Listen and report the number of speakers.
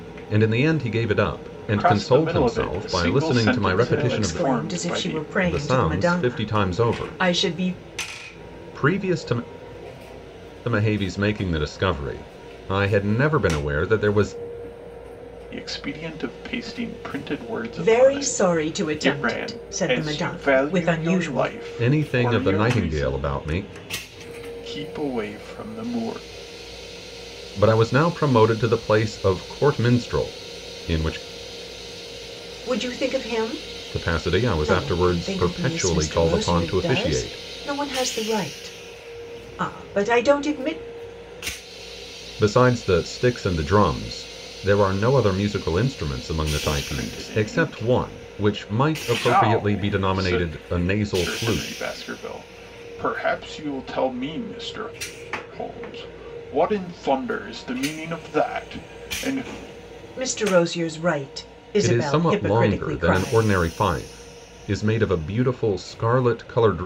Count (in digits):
3